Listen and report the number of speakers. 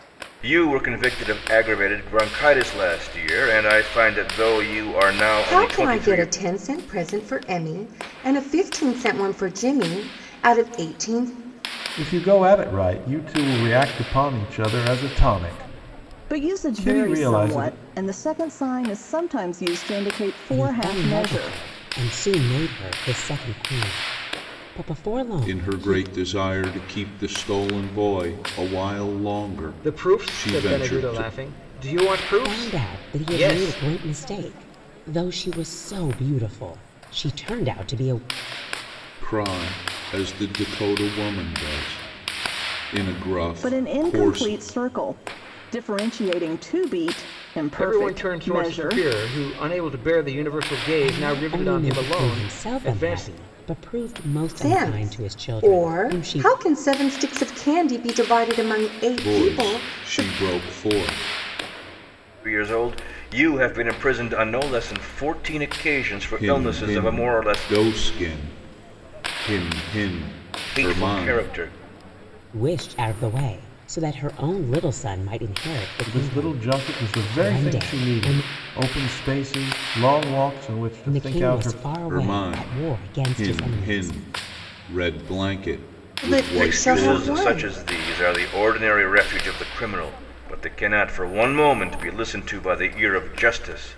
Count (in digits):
7